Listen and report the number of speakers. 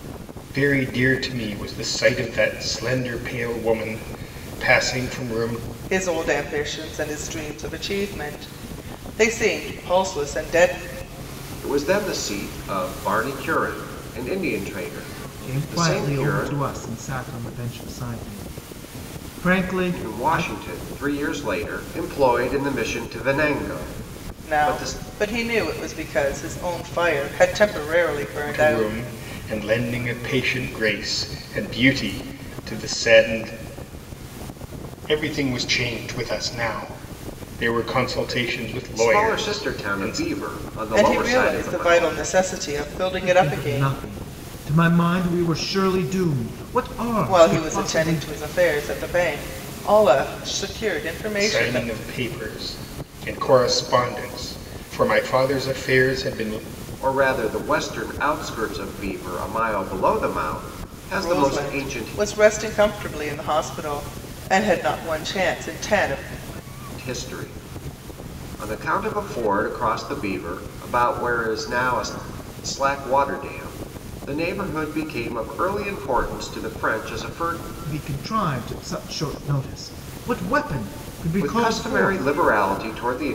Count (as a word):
four